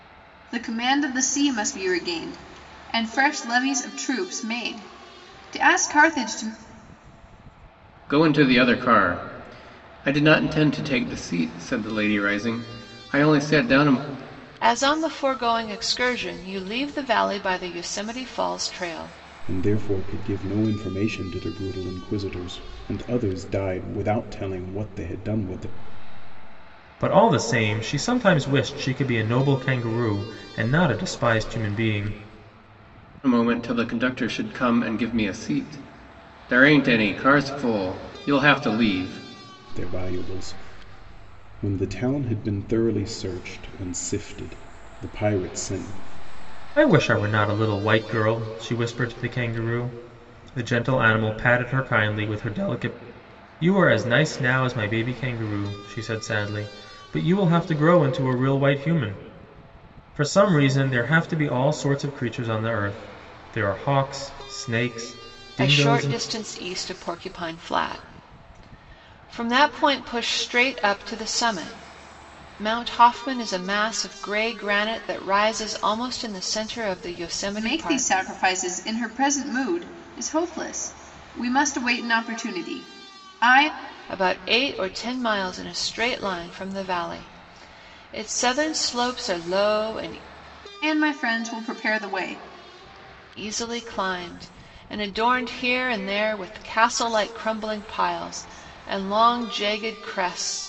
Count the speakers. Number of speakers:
5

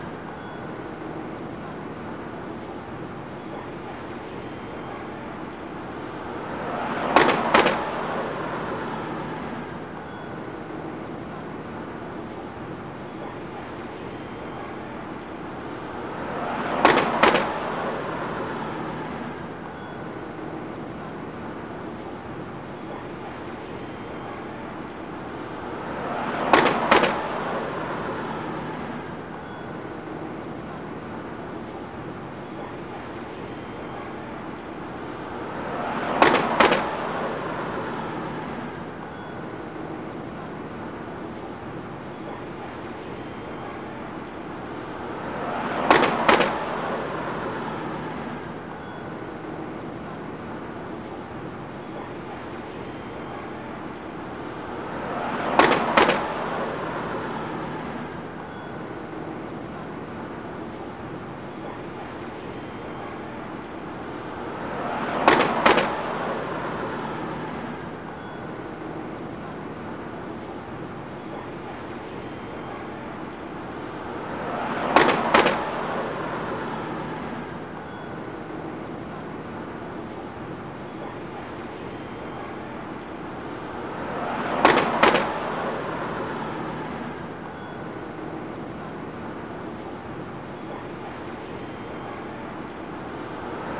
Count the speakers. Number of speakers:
0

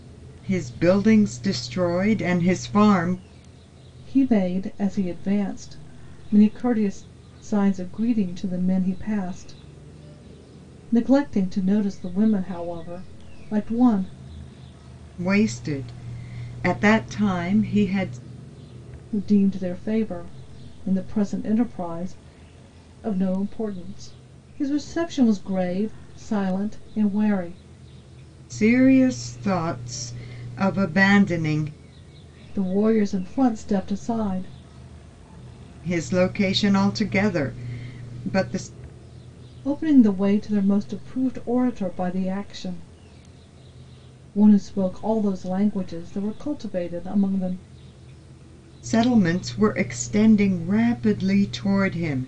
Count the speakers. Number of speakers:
2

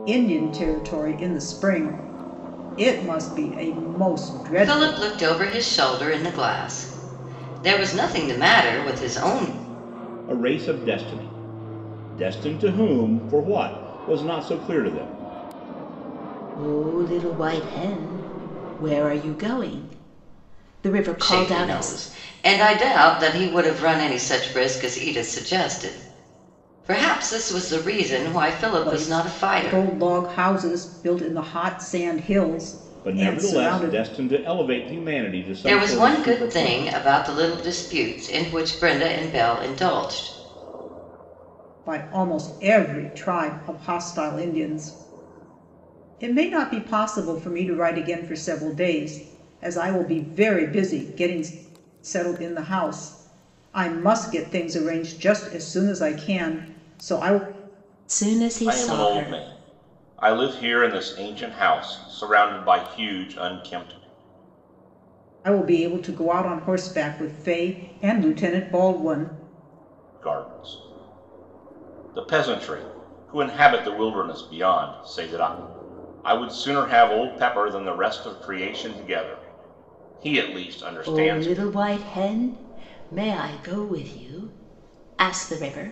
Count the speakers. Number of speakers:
4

